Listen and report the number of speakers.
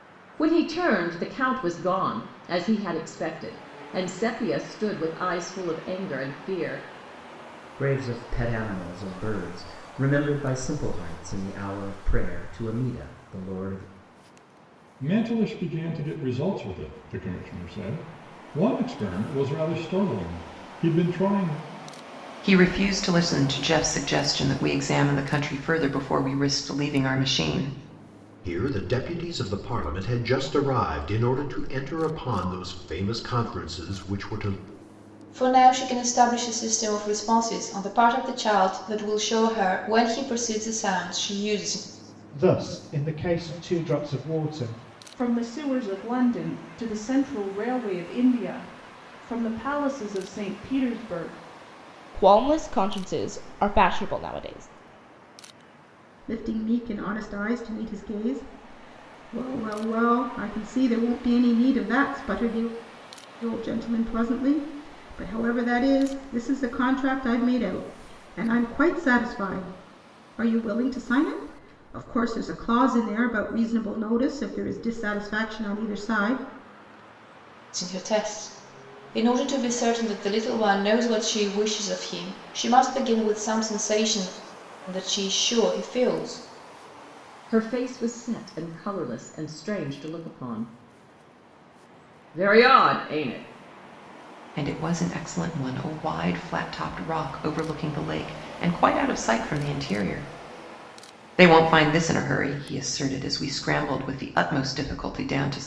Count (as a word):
ten